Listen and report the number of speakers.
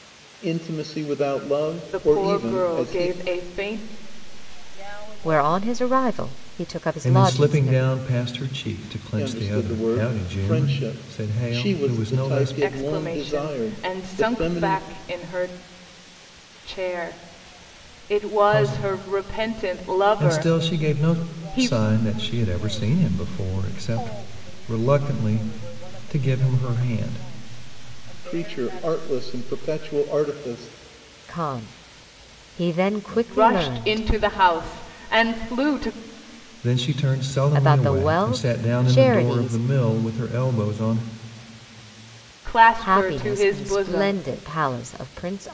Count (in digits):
5